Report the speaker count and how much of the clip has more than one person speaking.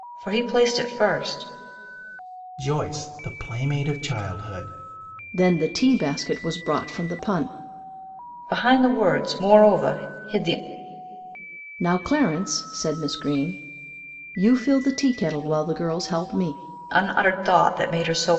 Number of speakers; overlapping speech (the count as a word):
three, no overlap